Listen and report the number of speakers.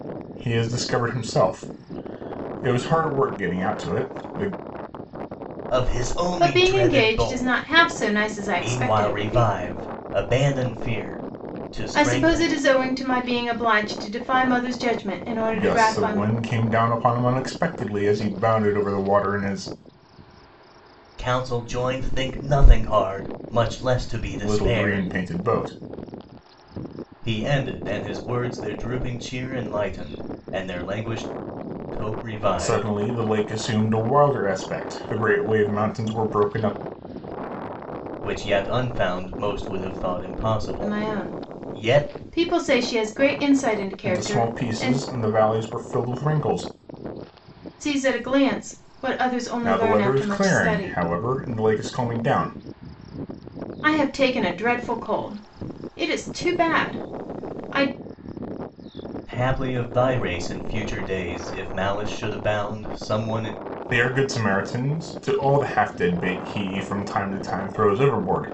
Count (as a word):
three